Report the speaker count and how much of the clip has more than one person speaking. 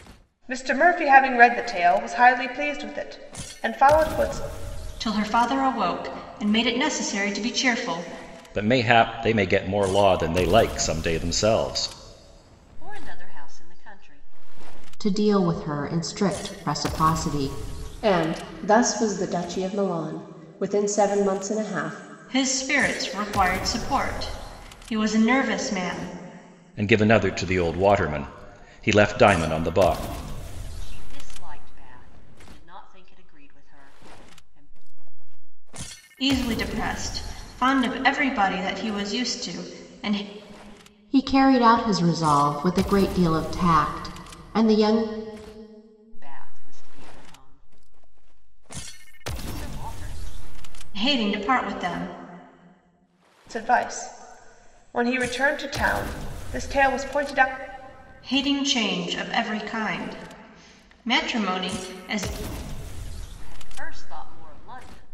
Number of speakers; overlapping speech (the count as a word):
six, no overlap